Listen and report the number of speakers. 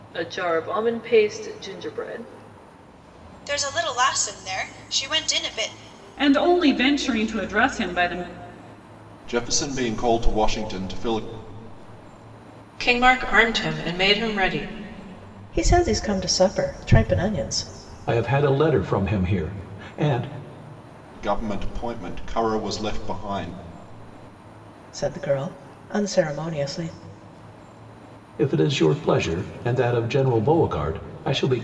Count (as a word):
seven